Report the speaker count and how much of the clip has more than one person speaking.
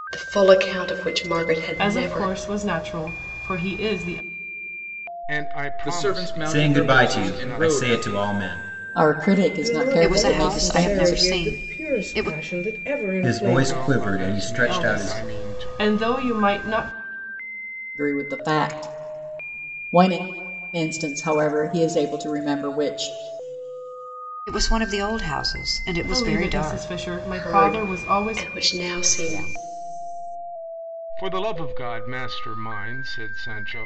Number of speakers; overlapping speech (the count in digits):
8, about 33%